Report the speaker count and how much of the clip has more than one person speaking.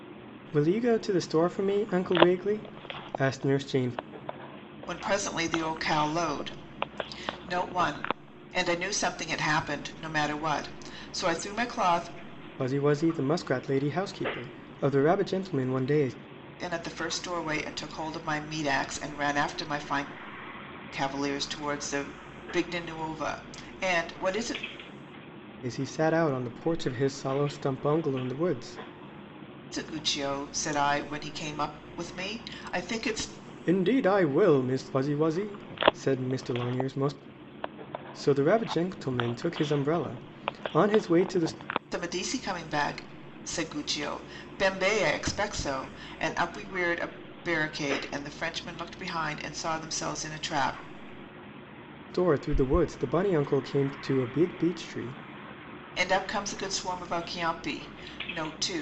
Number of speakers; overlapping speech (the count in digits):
2, no overlap